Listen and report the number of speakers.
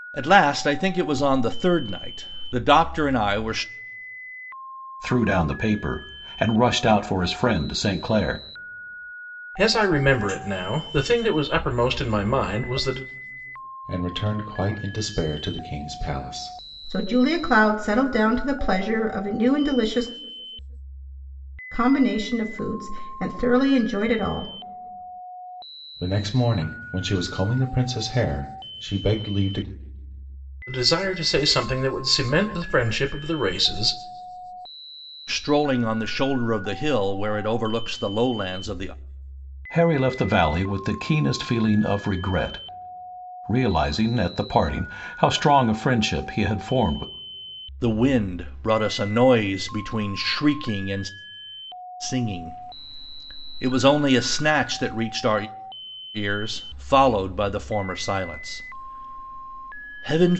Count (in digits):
5